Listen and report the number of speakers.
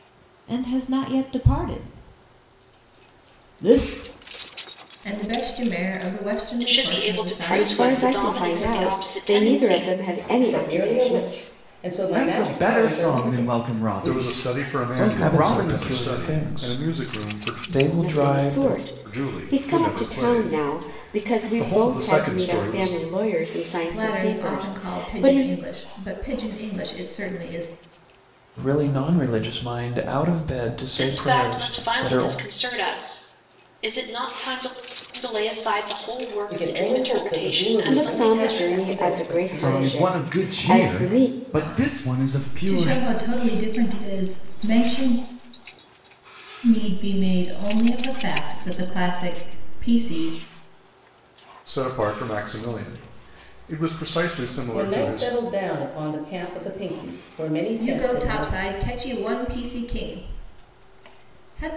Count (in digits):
8